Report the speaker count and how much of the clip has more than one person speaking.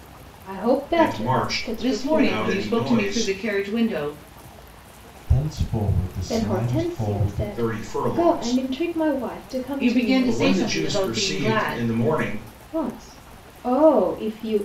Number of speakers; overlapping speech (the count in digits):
4, about 47%